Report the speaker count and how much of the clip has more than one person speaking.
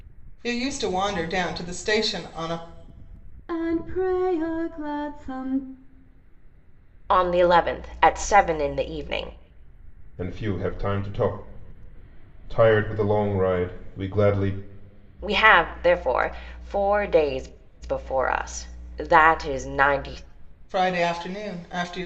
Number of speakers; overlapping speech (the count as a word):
four, no overlap